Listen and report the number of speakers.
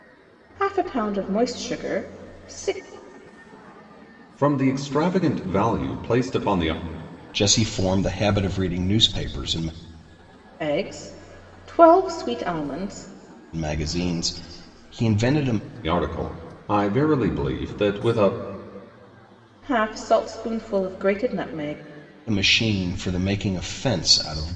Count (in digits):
3